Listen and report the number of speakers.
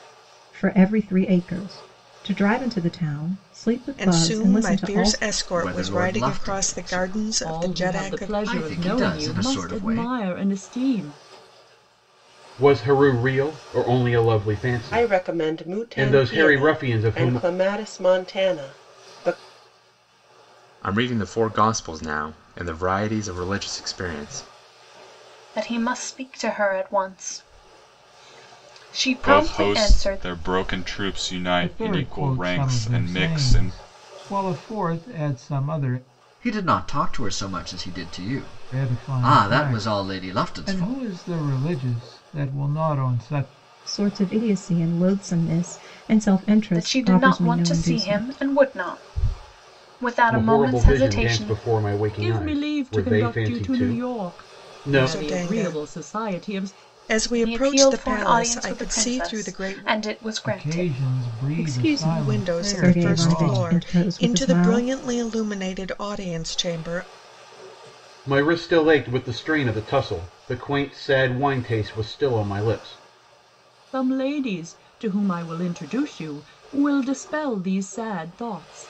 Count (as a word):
ten